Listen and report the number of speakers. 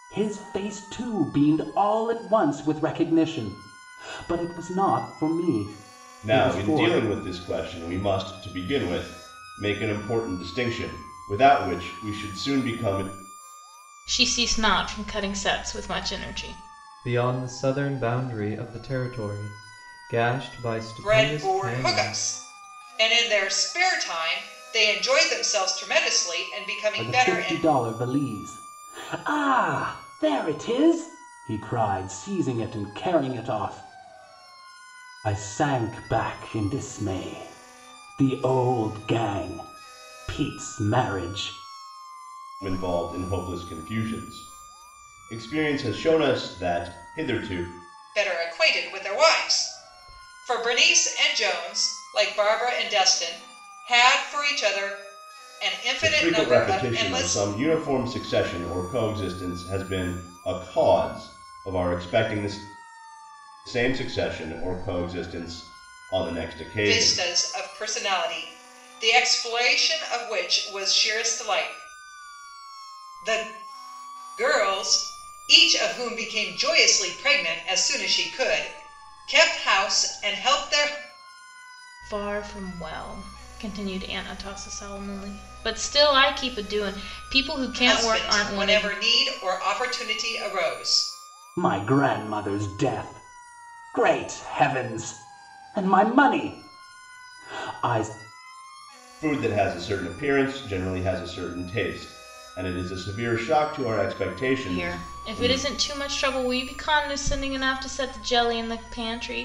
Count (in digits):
5